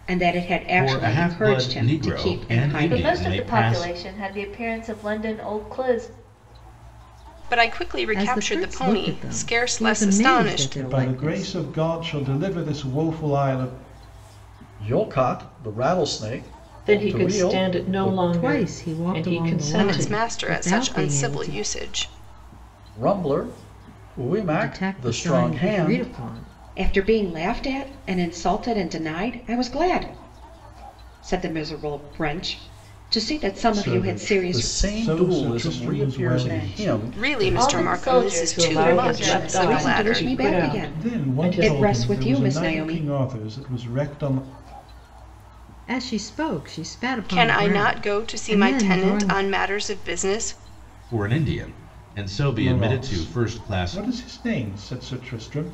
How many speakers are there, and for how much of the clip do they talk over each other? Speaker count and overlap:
eight, about 47%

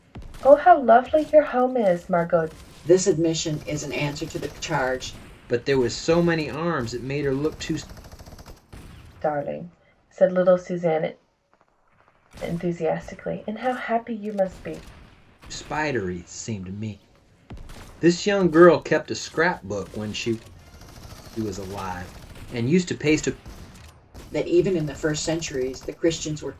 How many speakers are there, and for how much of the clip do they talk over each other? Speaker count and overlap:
three, no overlap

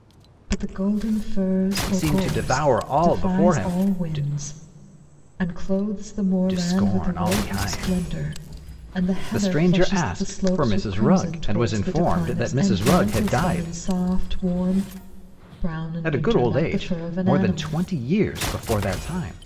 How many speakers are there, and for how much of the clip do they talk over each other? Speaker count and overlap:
two, about 52%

